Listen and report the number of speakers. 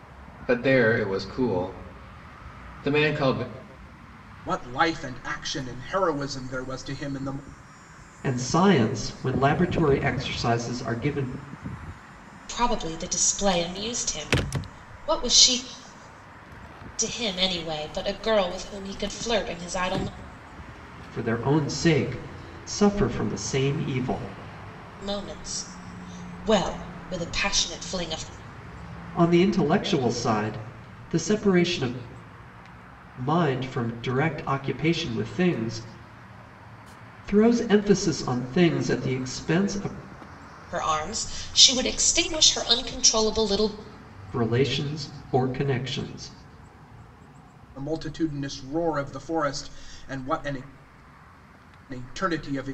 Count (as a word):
four